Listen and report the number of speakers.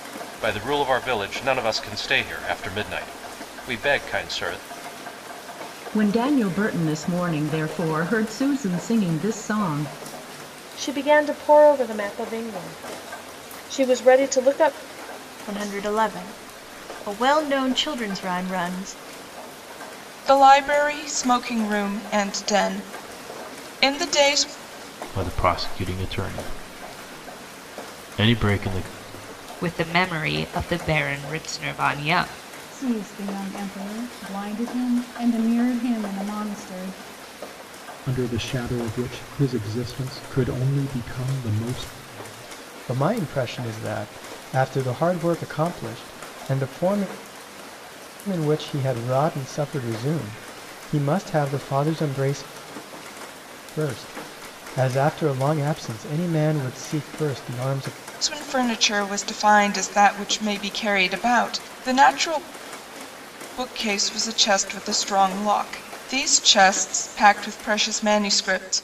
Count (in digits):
10